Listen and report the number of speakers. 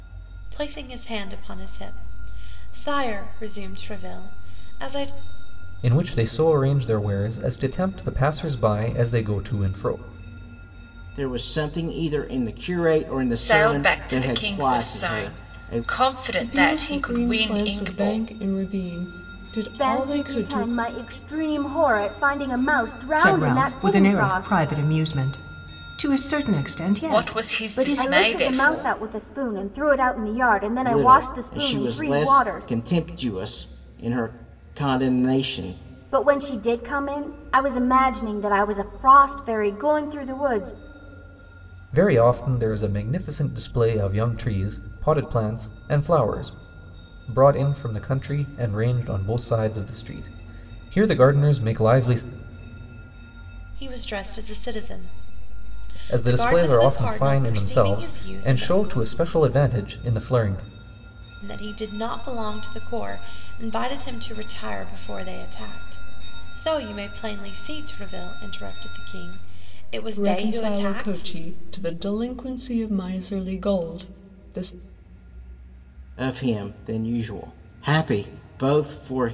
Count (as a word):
seven